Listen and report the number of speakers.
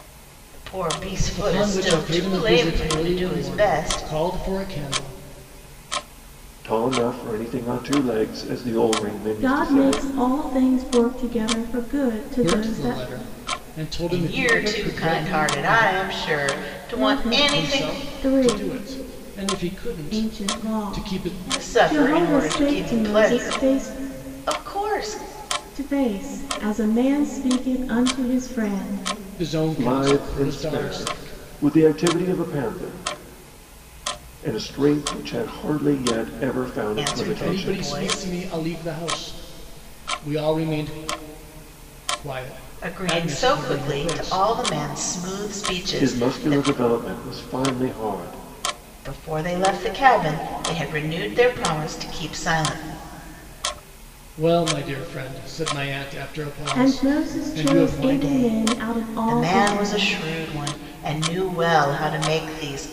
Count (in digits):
4